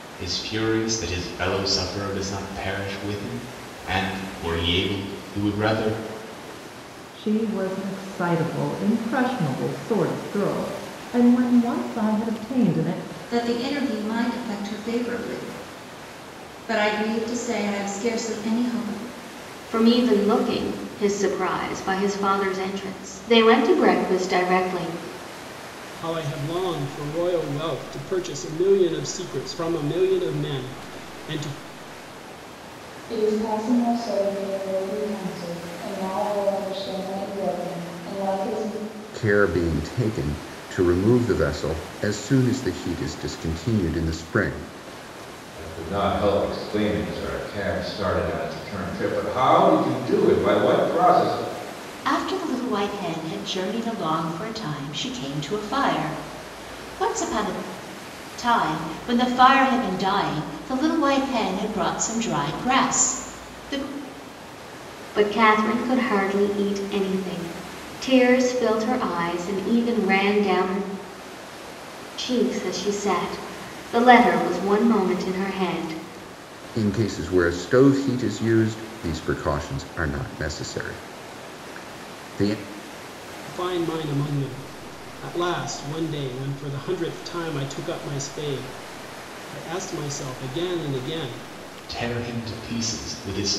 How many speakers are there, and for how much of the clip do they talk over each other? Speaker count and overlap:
nine, no overlap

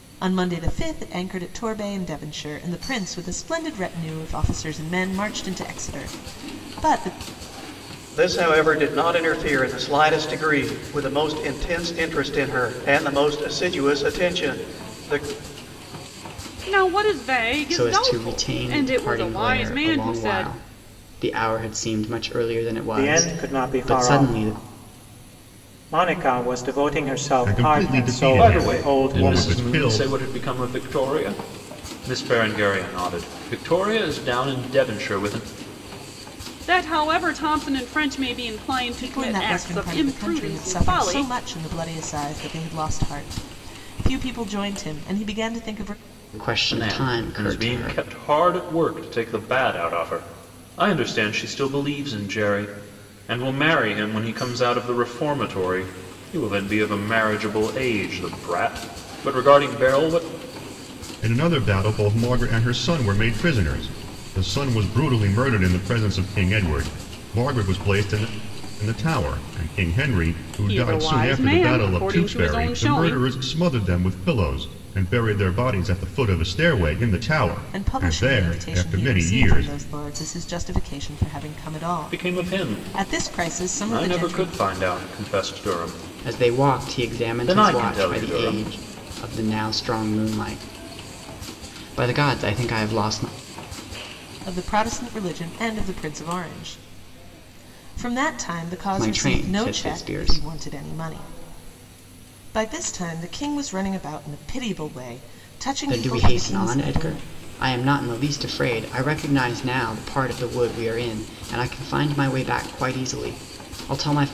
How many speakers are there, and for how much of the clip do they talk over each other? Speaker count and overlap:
seven, about 21%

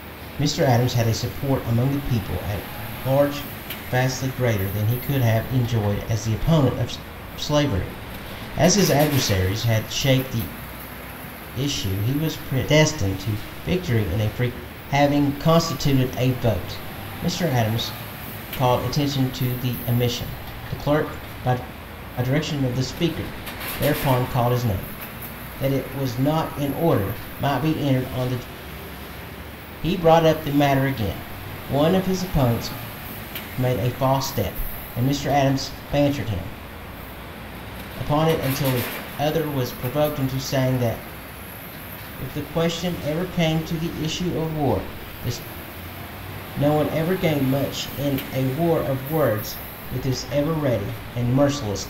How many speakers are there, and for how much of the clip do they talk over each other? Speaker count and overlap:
one, no overlap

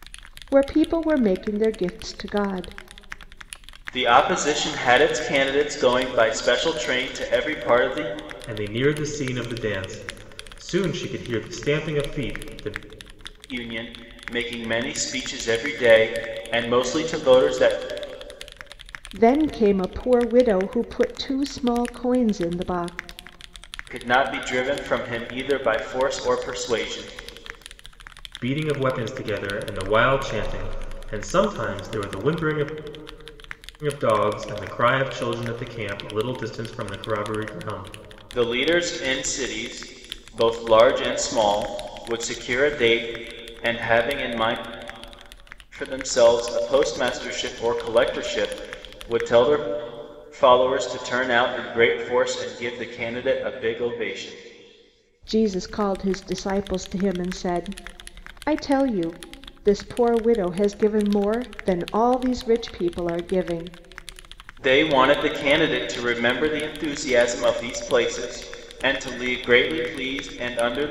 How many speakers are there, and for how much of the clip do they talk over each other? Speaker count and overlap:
three, no overlap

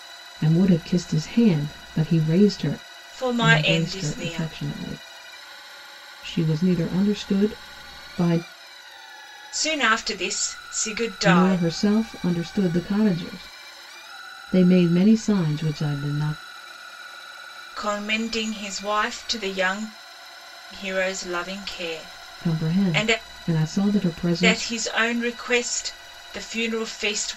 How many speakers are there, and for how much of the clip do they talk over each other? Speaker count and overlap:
two, about 10%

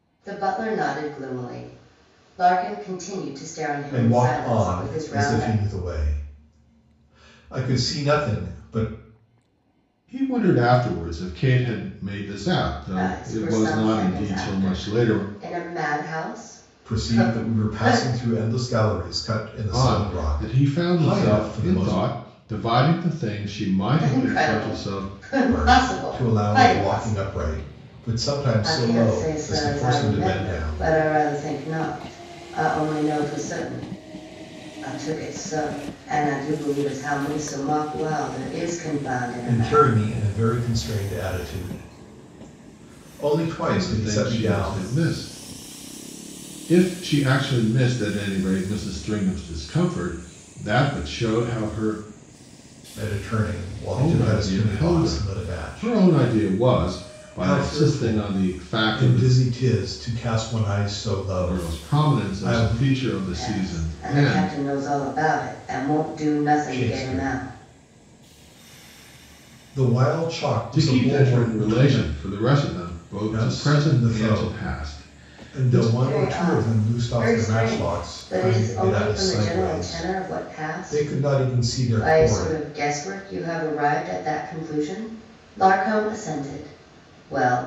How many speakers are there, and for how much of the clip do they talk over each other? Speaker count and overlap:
three, about 36%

